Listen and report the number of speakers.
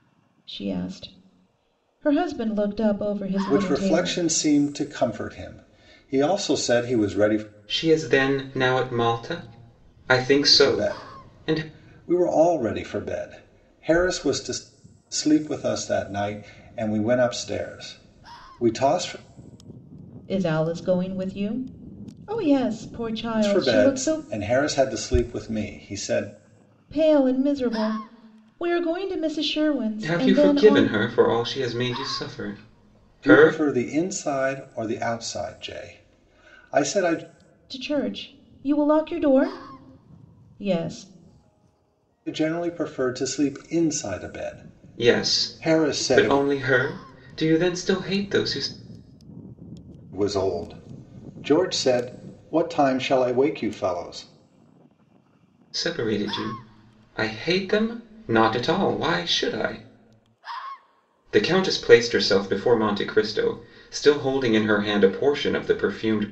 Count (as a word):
three